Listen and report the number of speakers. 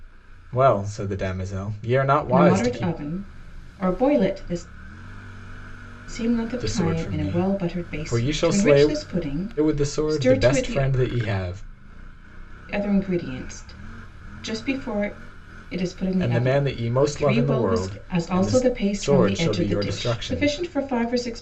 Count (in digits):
2